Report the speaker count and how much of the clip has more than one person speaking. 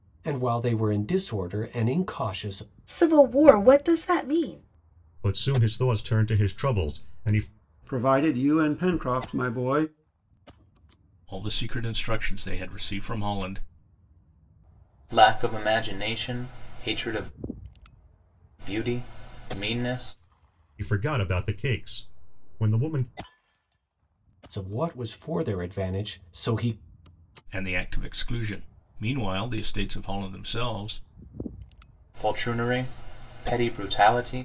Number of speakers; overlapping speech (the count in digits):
6, no overlap